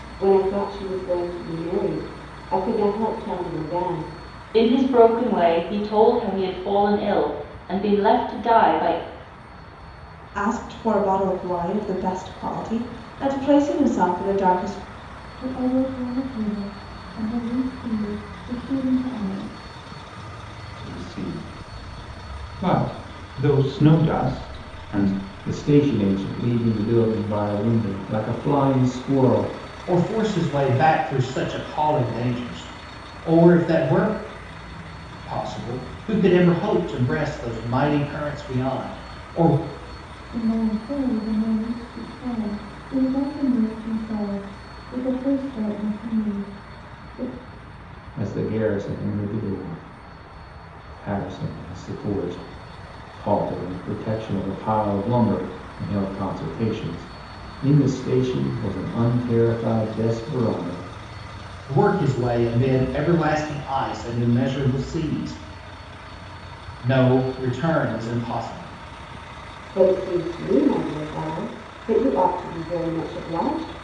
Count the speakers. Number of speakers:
7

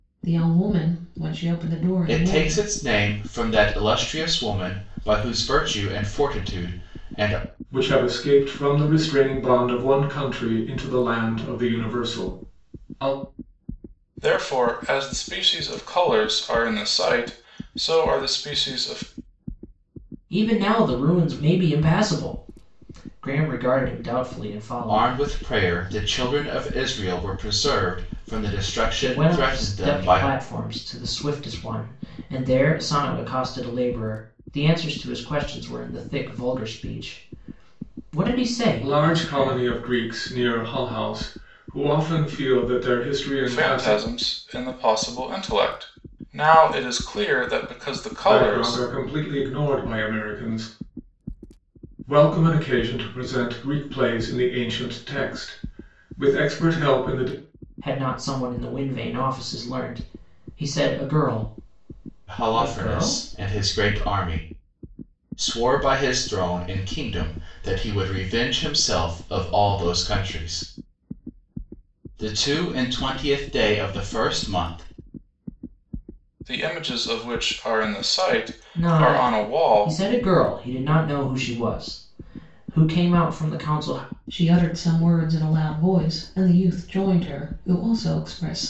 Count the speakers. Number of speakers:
5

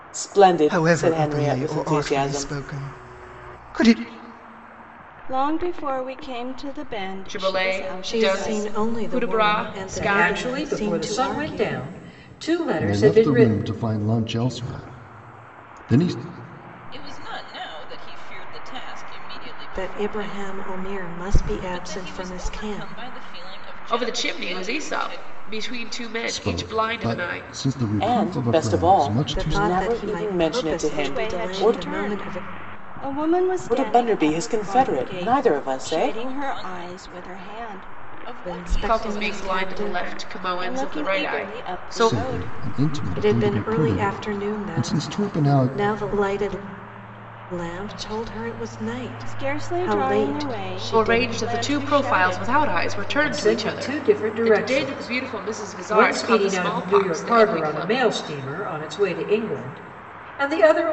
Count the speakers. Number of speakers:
8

